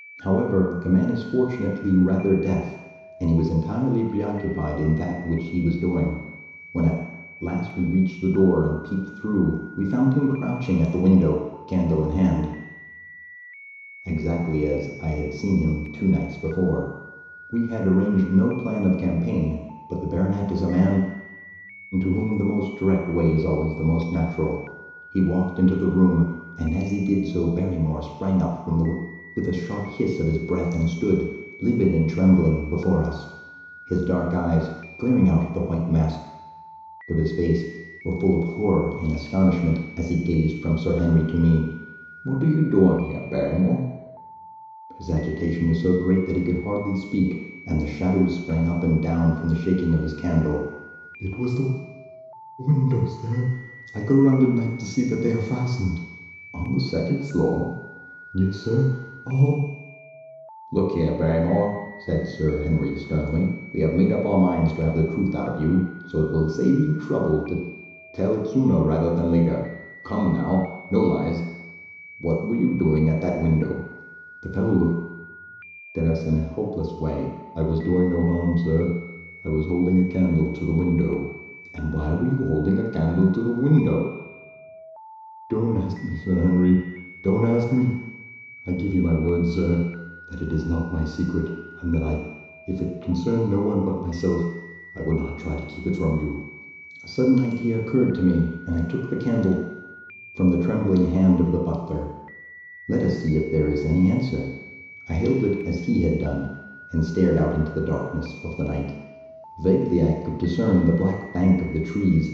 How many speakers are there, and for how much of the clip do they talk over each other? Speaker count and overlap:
1, no overlap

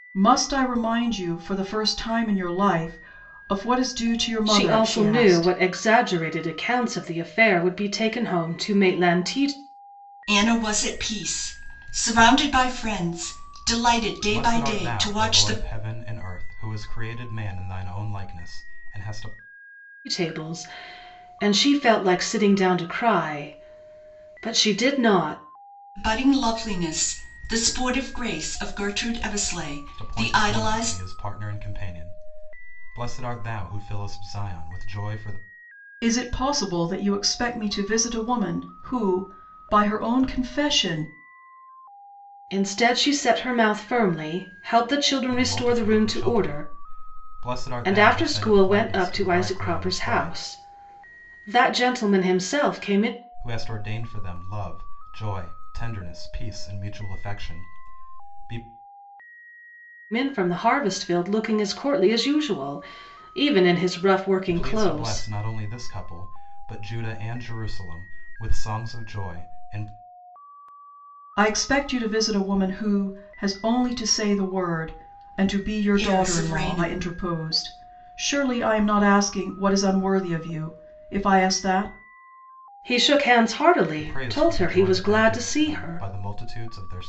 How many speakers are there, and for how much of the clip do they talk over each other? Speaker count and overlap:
4, about 13%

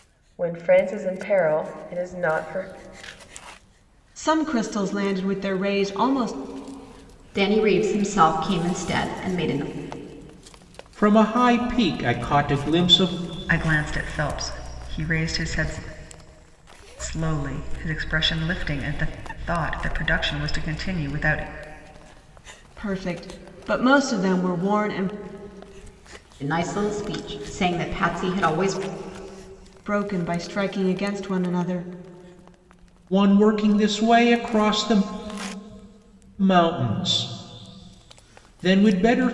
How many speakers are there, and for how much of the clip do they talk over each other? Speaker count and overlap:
5, no overlap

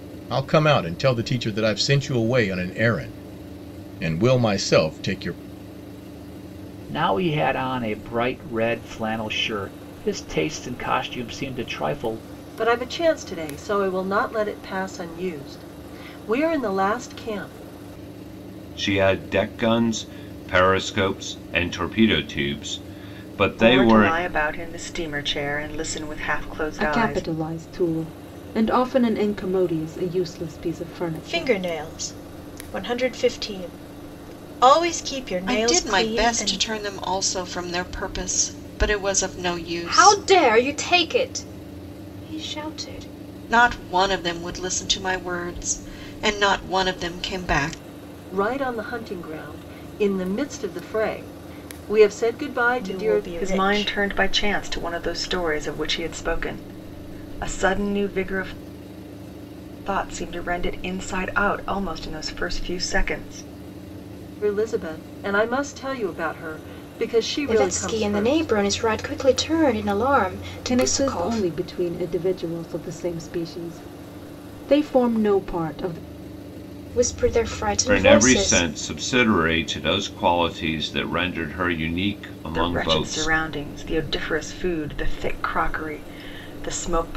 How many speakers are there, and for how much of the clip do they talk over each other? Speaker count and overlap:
9, about 9%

